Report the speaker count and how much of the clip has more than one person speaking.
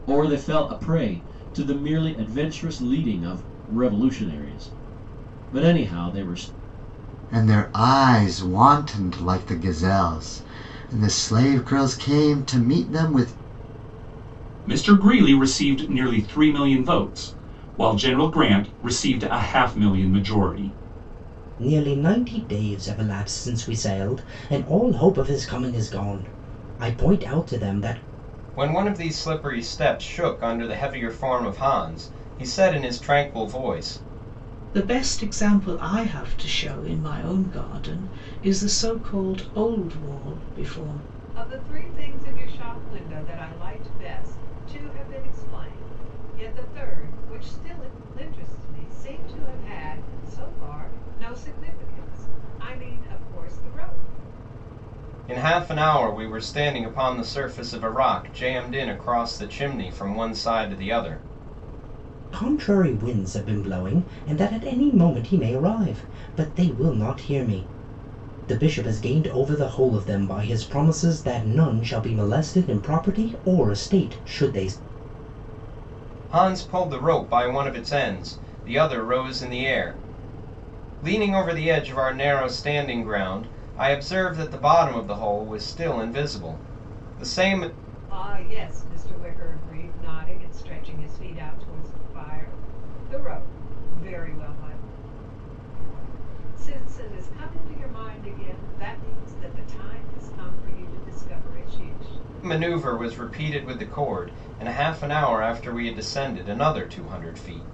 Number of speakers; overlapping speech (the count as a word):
seven, no overlap